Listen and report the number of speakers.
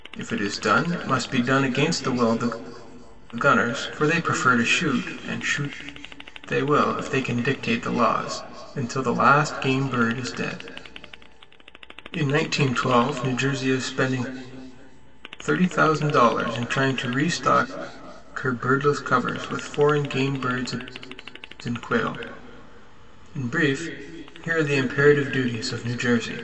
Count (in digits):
1